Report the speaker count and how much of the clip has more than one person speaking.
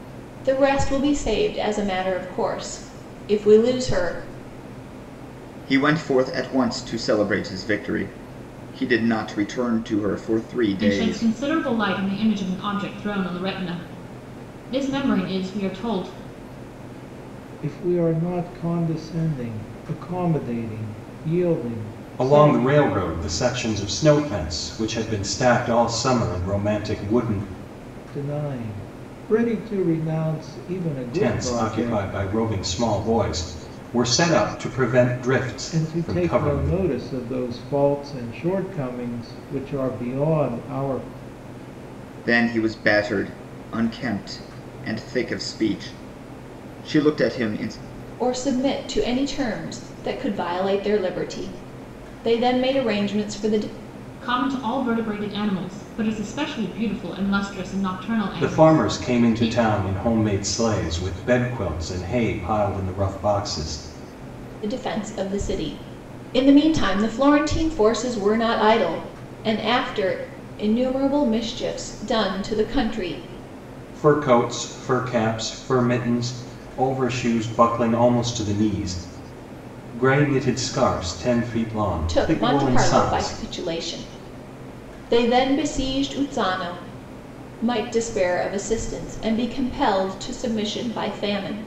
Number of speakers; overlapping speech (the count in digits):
5, about 6%